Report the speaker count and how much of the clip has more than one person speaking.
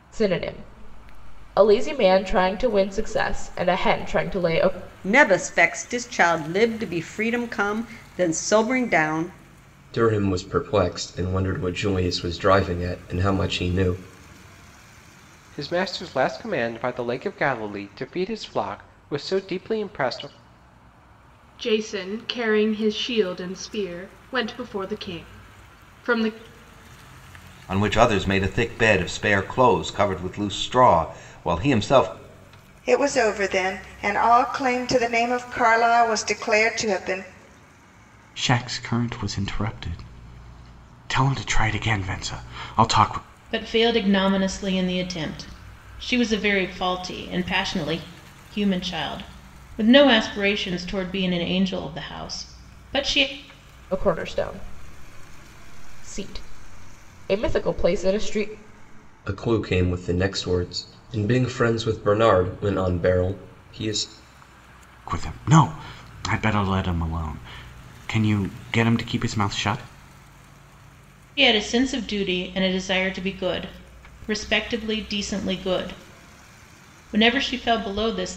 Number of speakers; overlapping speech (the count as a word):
nine, no overlap